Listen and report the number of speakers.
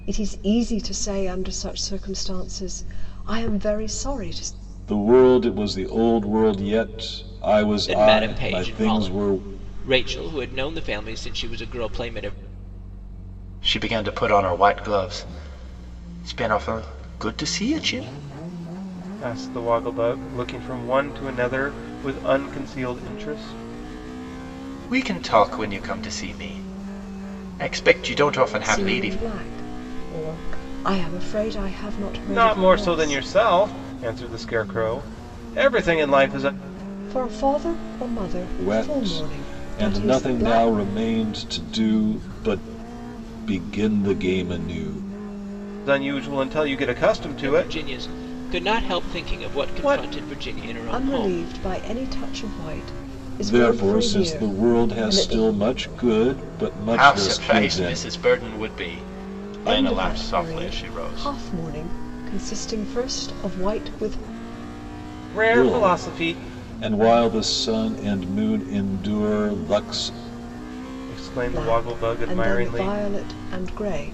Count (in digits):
5